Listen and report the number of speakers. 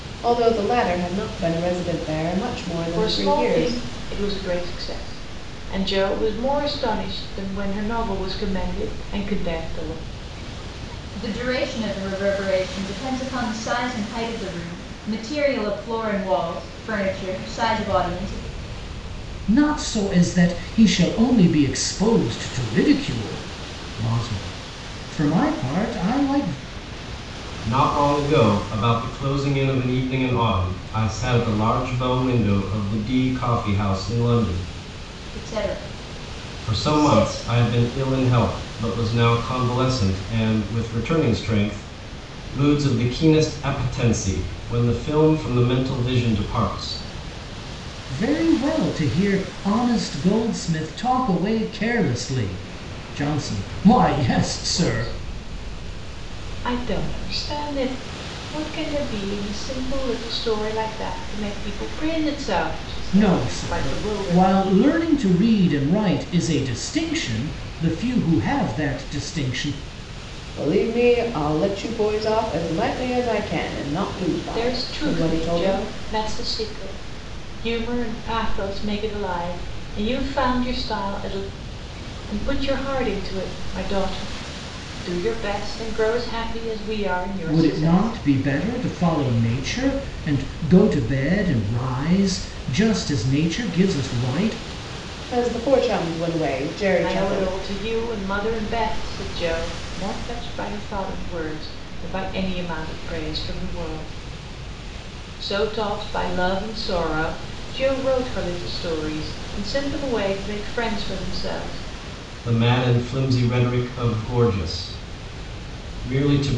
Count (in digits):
5